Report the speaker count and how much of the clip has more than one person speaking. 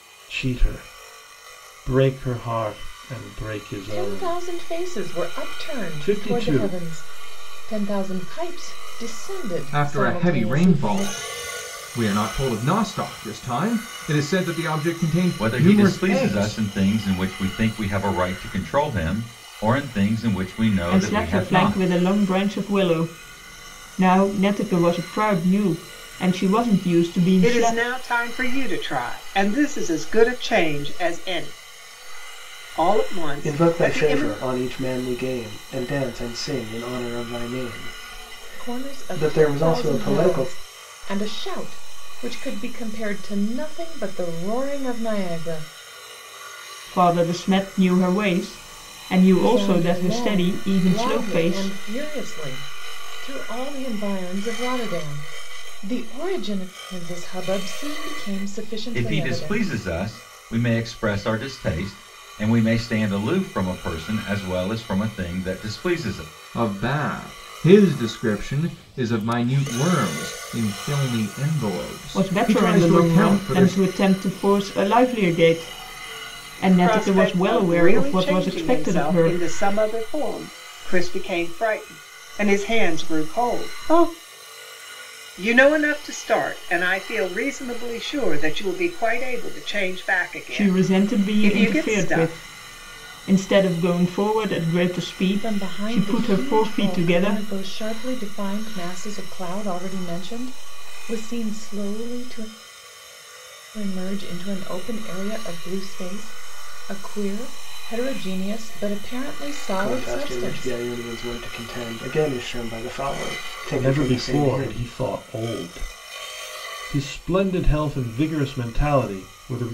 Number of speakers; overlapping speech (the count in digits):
7, about 20%